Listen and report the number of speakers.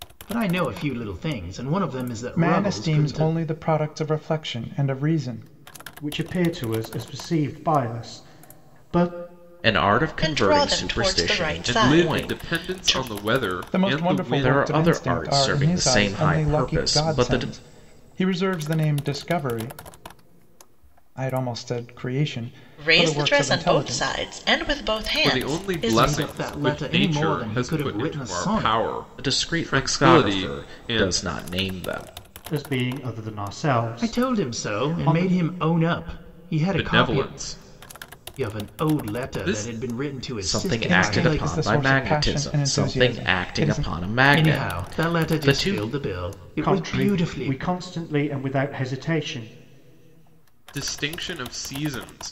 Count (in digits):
6